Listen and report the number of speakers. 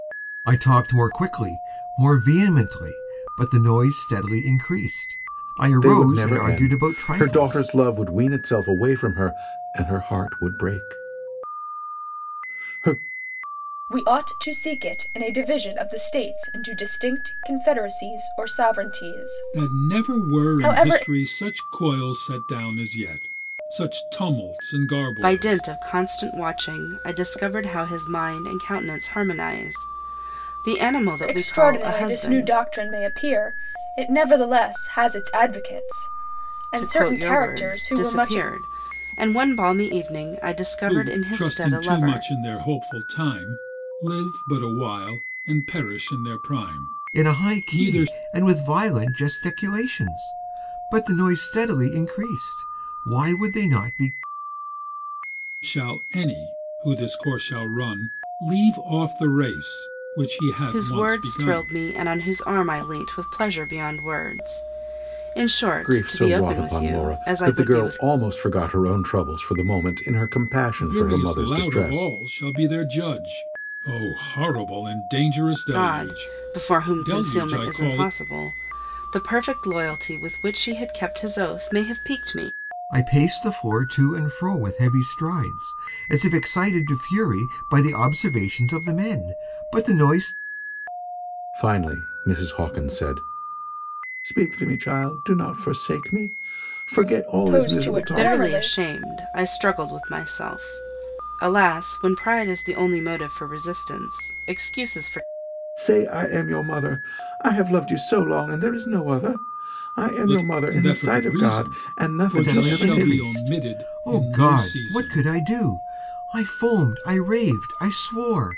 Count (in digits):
5